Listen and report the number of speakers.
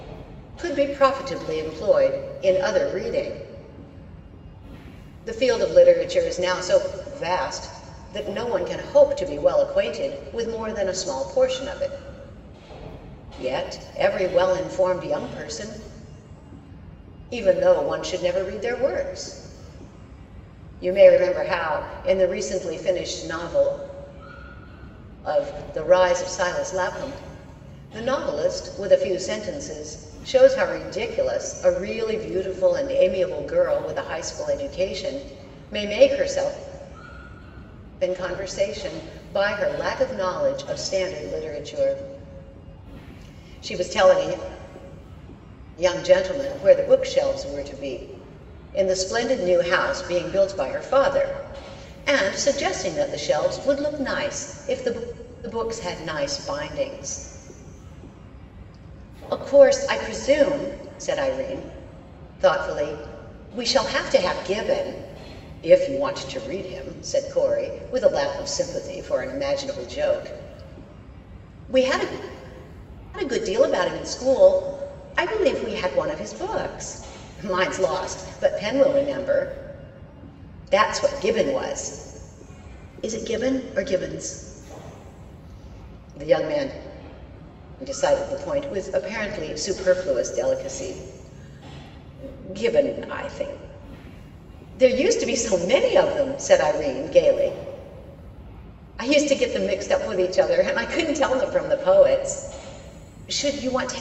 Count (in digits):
1